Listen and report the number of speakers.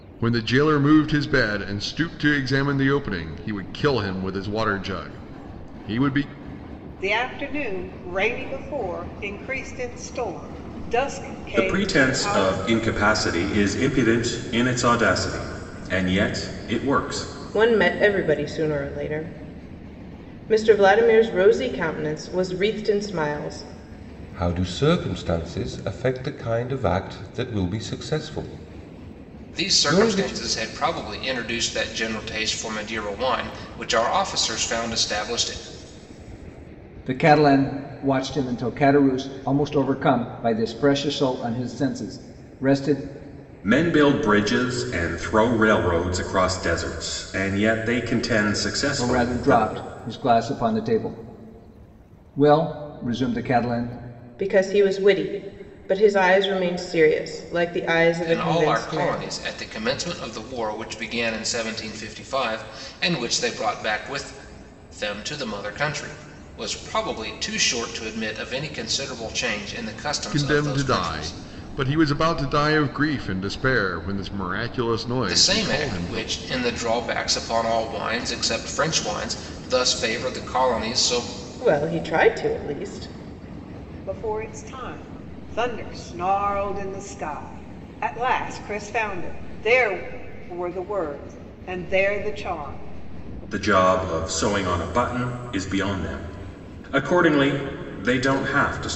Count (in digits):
7